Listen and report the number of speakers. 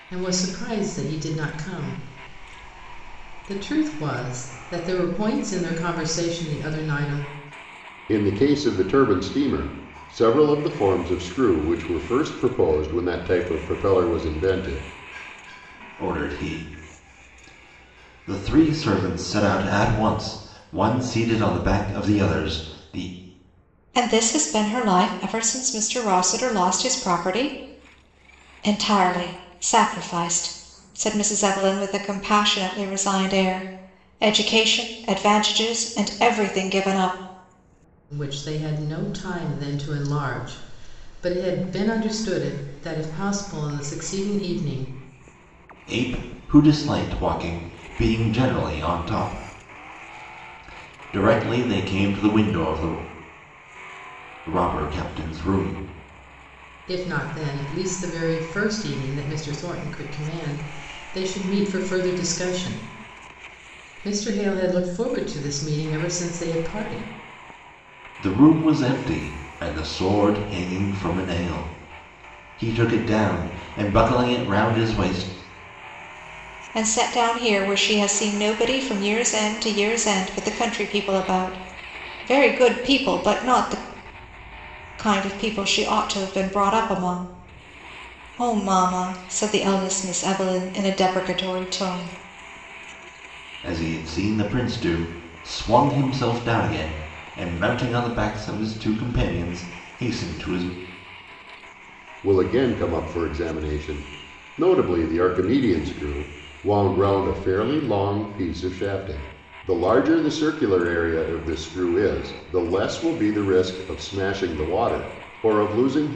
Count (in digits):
4